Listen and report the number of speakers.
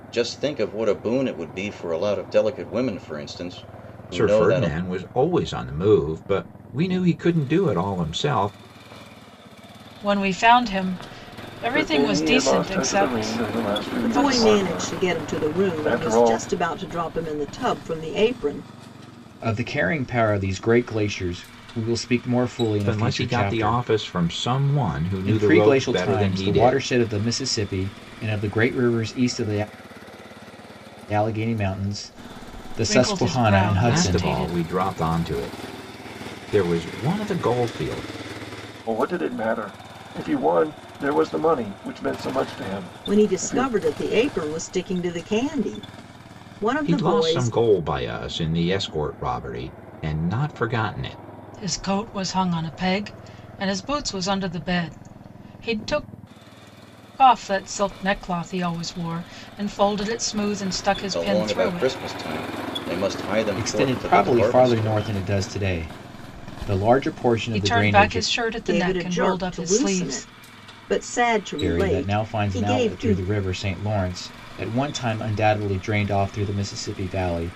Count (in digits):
6